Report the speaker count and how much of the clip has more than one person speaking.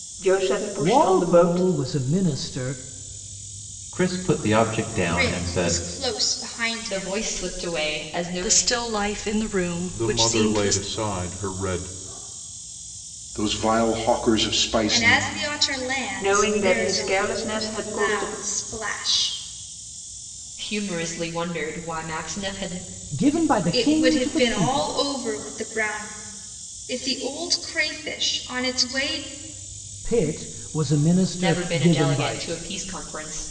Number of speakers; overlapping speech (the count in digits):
8, about 23%